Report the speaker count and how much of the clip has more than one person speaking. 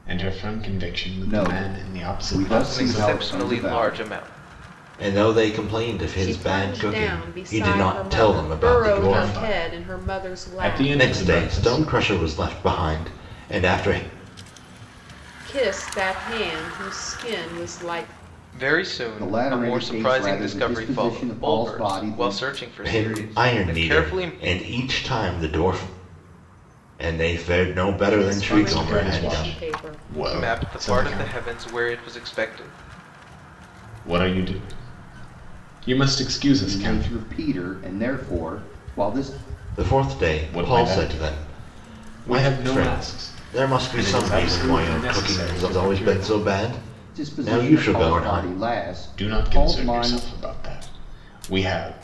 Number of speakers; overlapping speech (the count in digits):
5, about 48%